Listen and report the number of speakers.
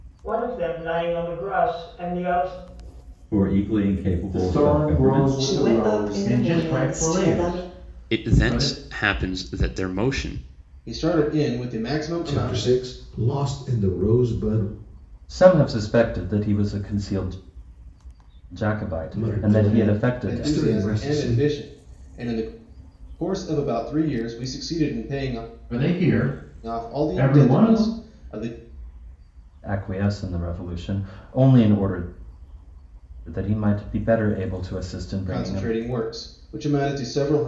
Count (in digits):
9